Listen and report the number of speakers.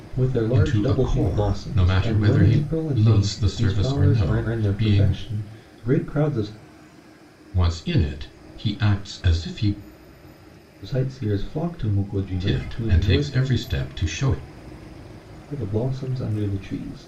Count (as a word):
two